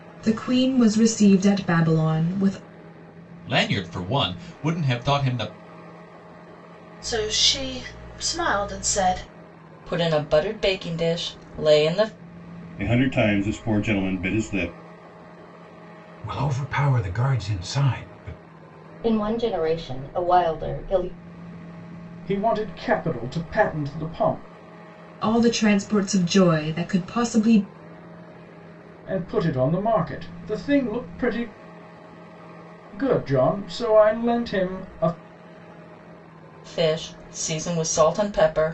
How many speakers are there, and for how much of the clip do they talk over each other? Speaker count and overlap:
eight, no overlap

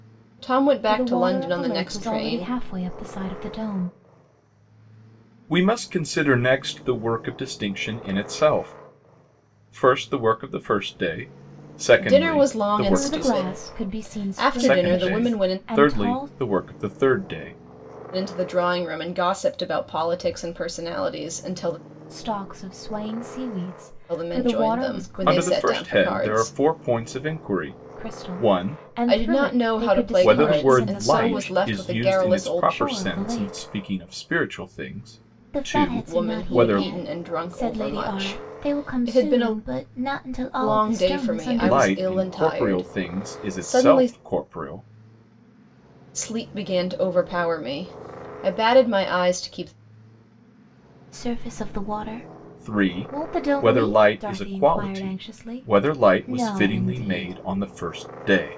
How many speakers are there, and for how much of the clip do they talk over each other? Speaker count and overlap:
three, about 45%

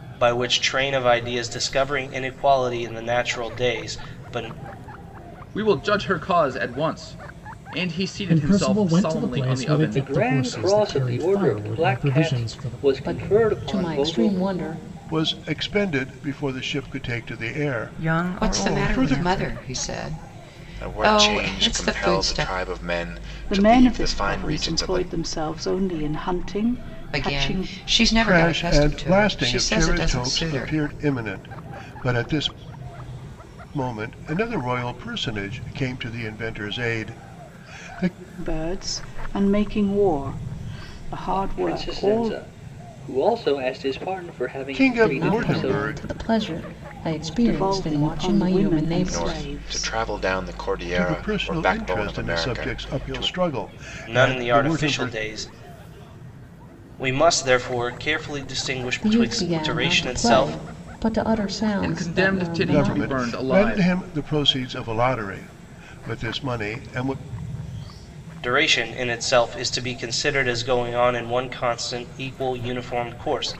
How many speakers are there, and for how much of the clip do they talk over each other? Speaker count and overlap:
ten, about 36%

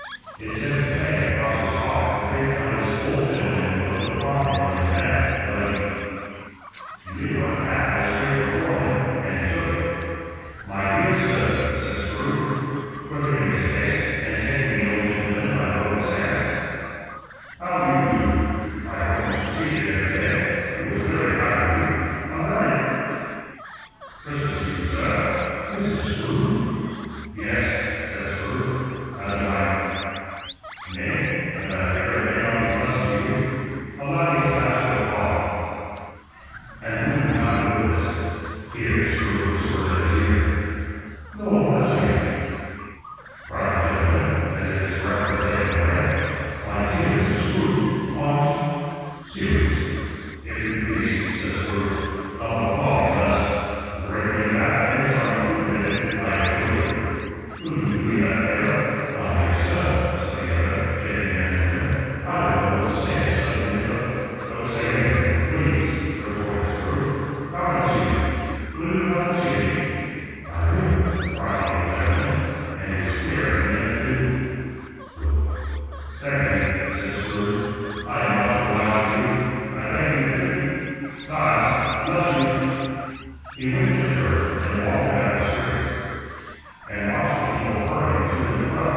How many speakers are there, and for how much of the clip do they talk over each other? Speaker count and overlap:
one, no overlap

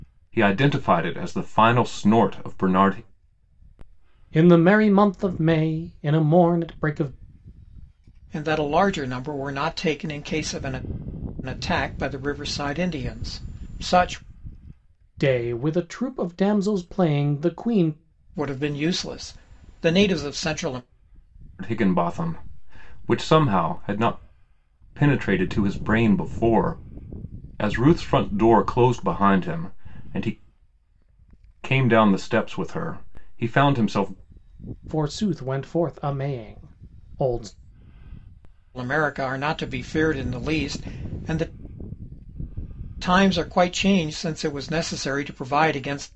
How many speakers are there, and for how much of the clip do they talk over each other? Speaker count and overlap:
three, no overlap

